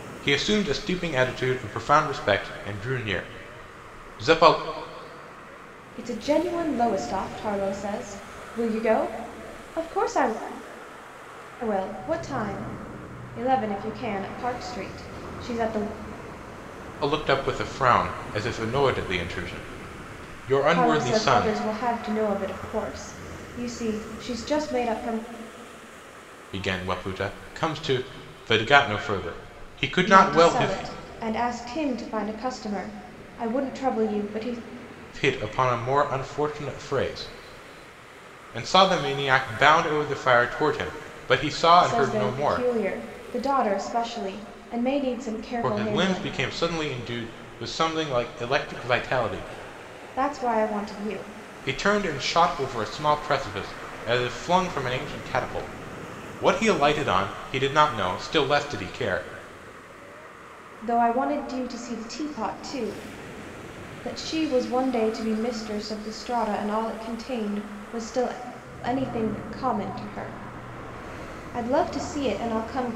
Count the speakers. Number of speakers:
2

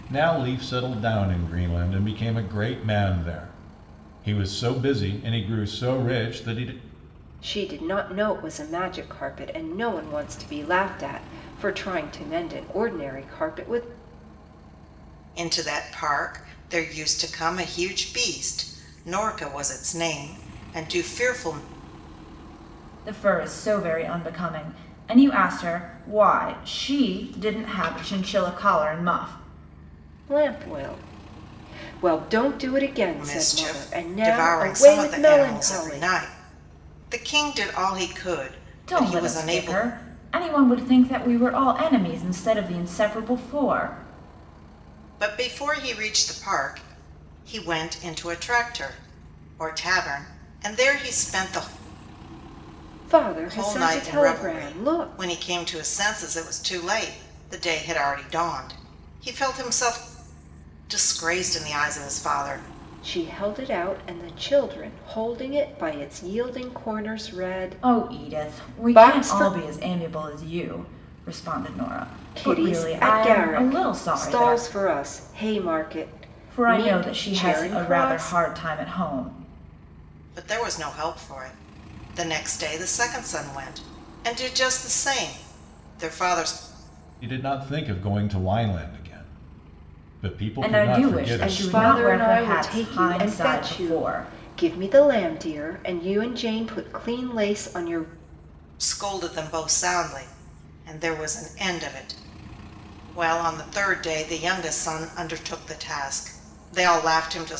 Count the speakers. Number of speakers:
4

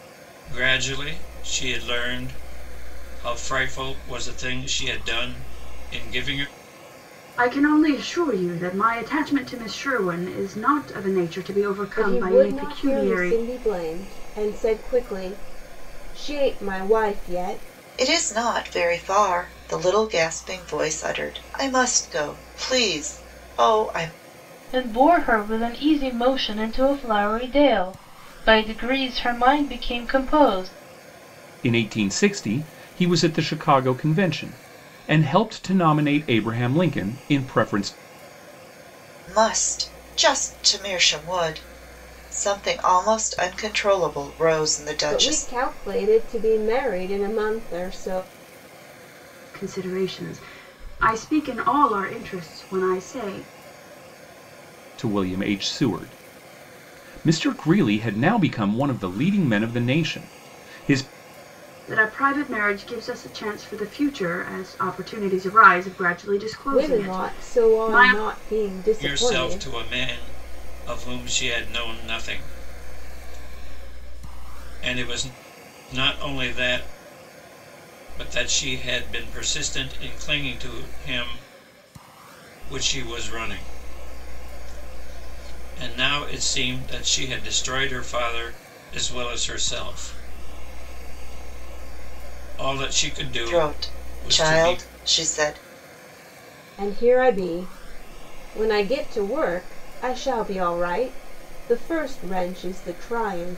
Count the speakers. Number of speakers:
6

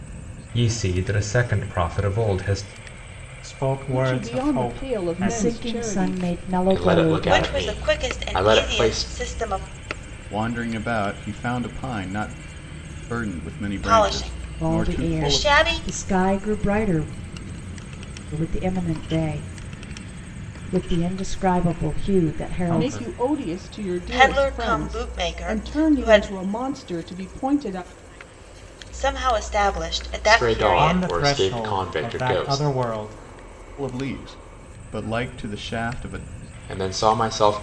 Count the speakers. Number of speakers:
7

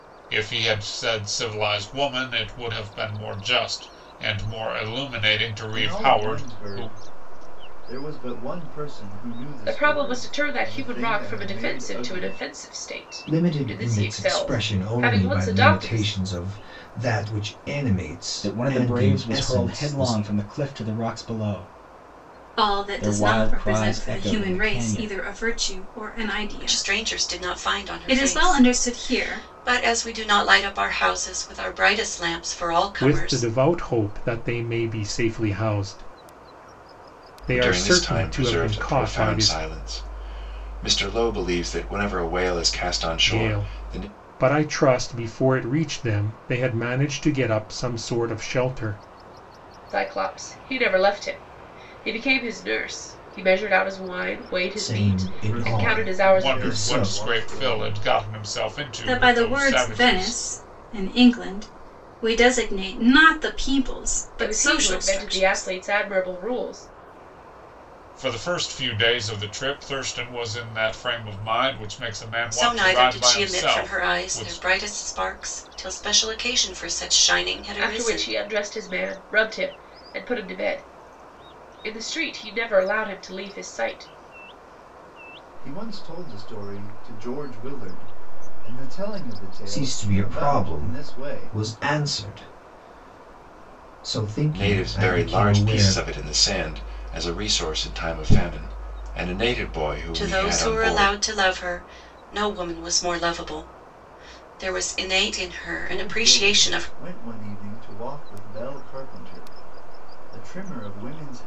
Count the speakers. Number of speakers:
9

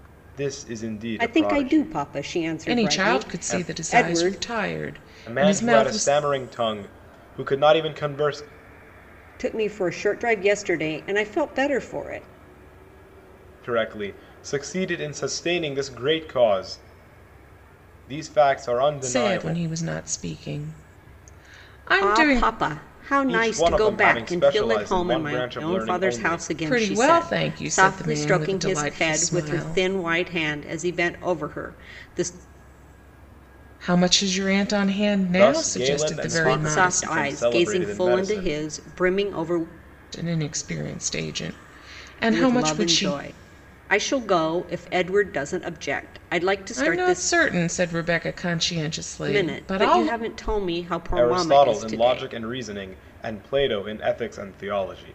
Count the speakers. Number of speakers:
3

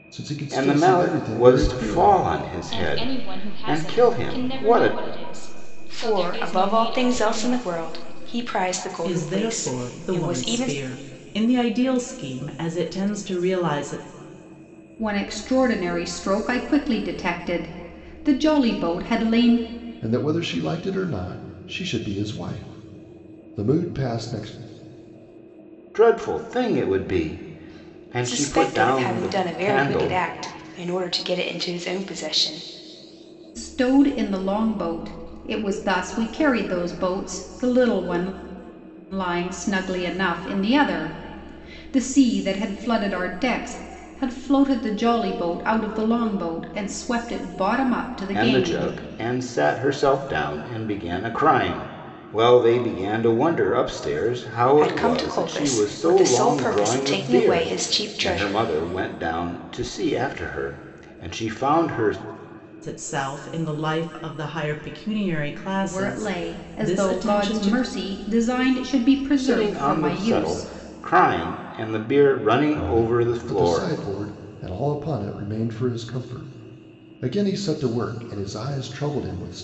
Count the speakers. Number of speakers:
6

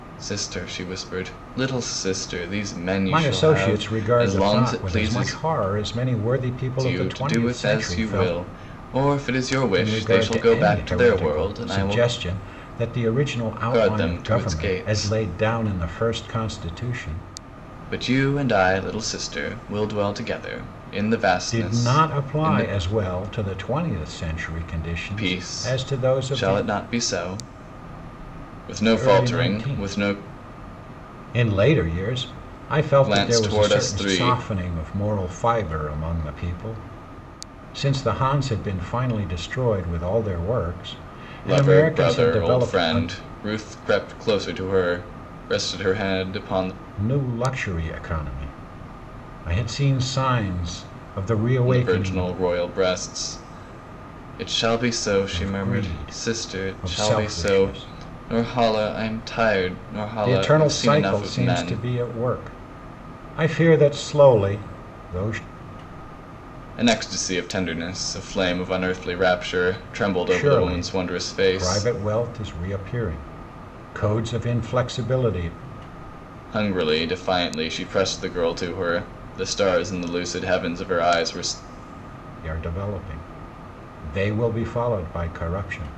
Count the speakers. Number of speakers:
2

